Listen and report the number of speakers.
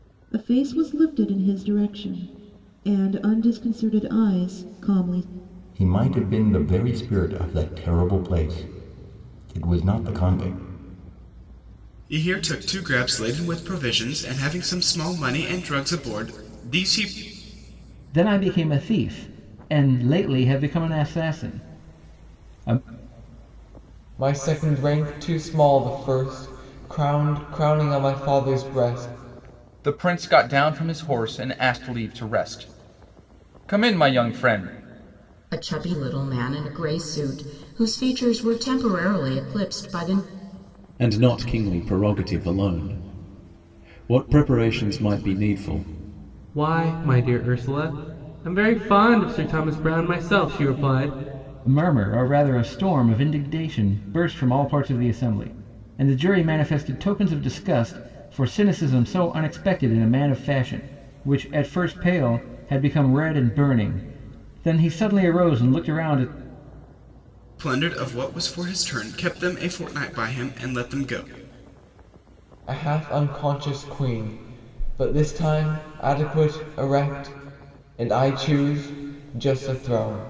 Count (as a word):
nine